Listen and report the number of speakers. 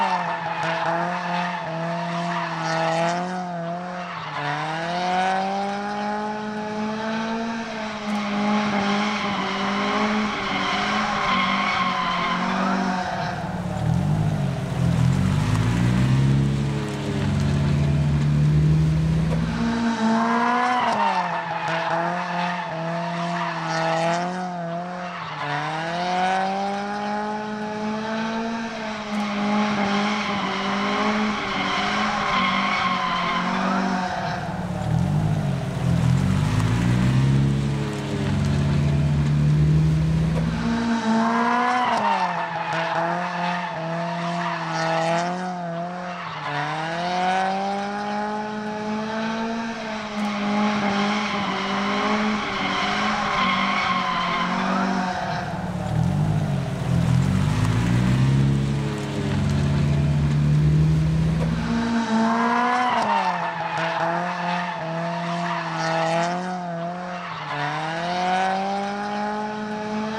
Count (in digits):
0